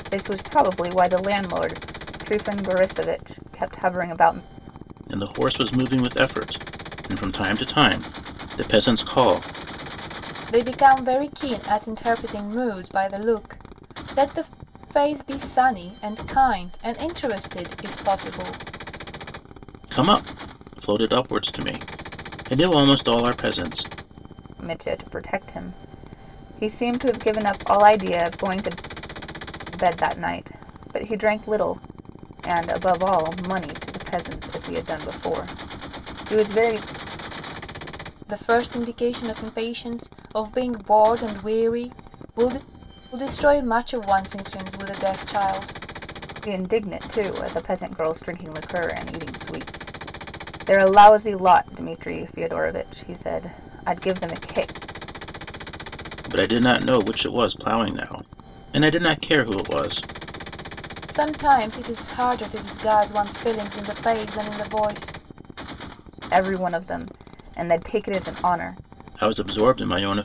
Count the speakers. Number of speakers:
3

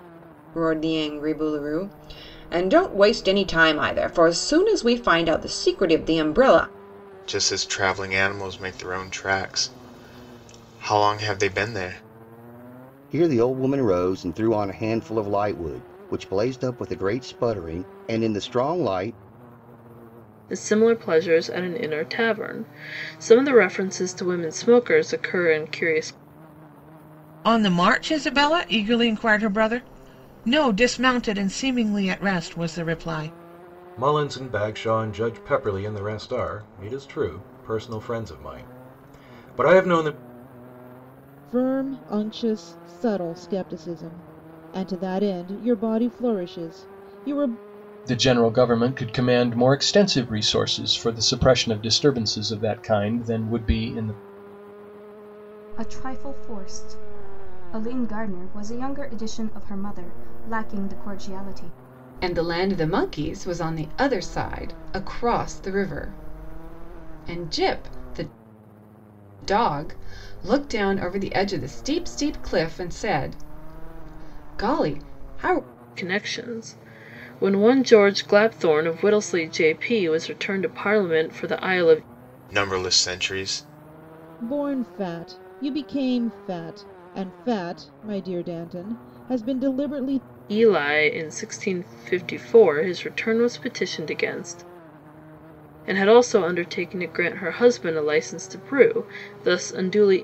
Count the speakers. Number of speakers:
10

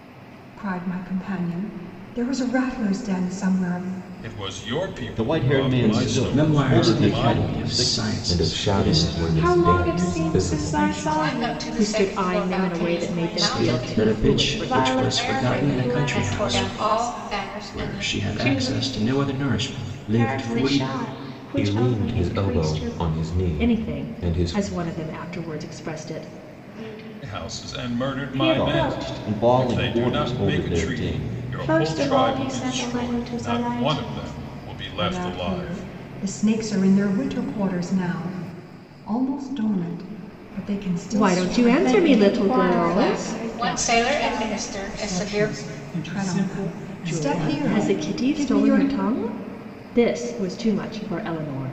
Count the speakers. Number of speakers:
9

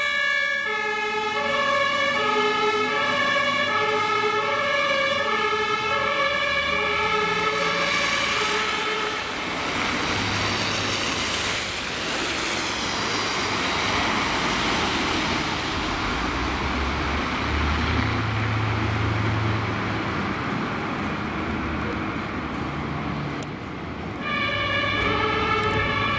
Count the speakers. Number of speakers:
0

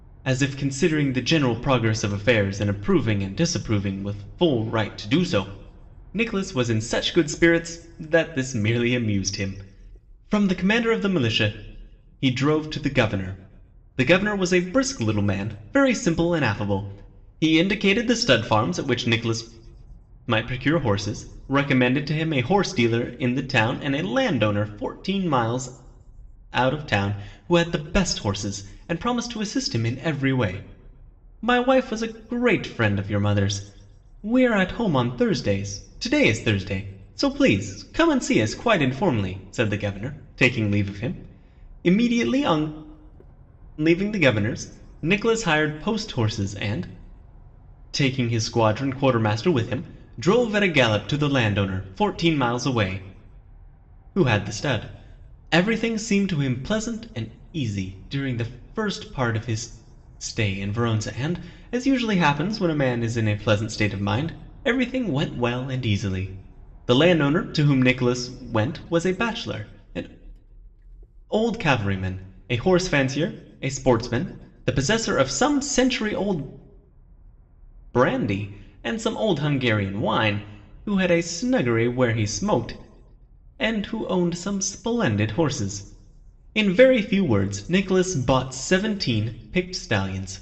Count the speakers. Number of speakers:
1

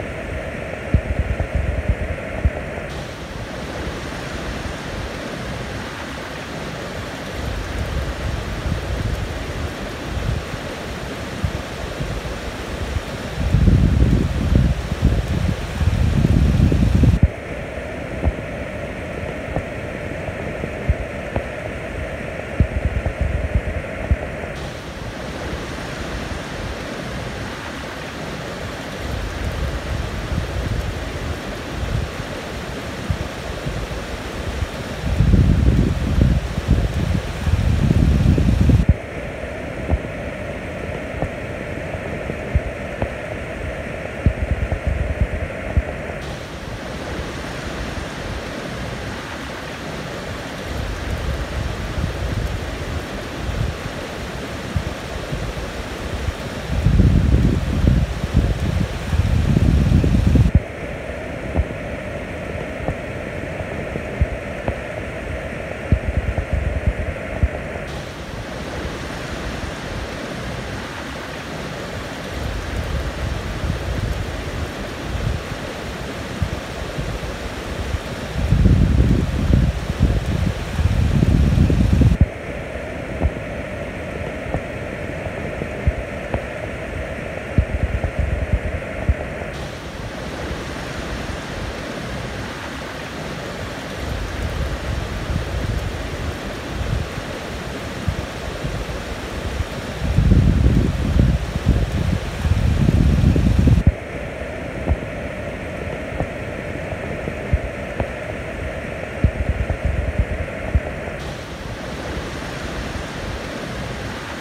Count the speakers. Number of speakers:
0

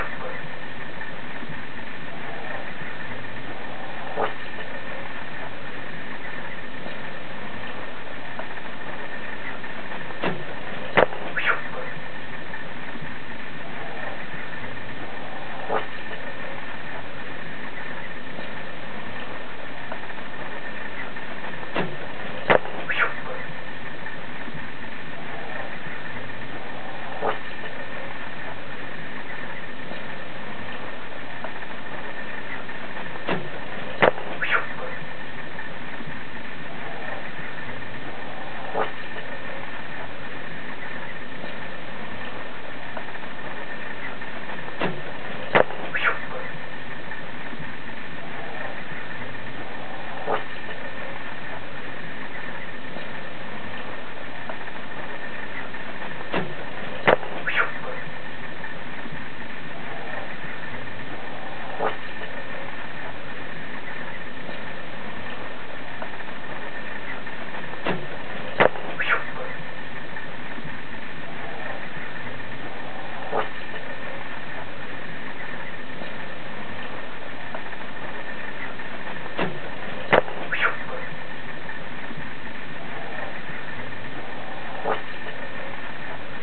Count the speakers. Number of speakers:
0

